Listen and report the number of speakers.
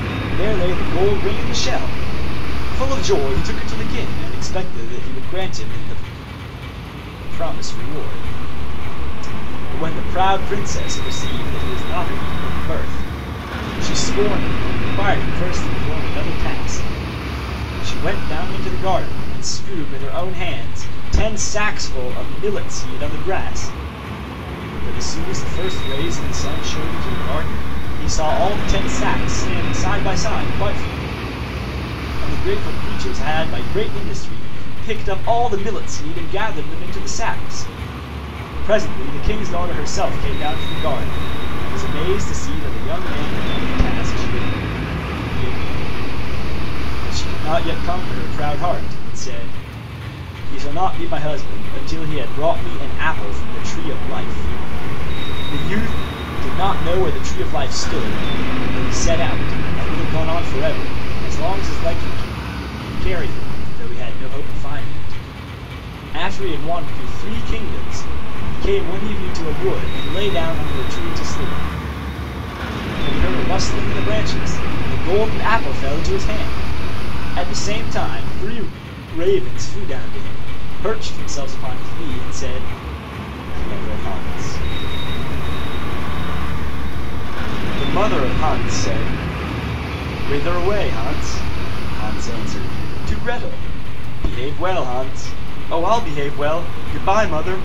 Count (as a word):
one